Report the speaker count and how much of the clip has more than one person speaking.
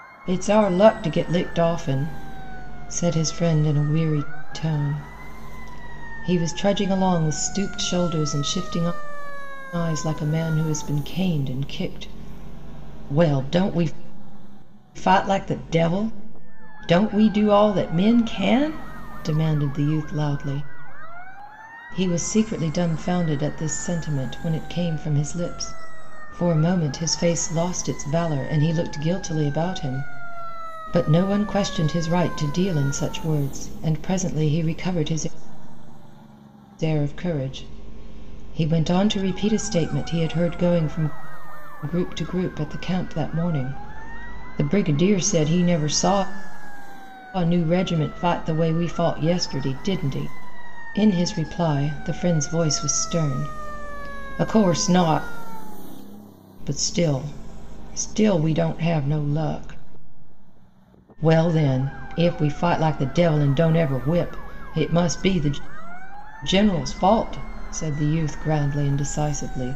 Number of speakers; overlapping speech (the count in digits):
1, no overlap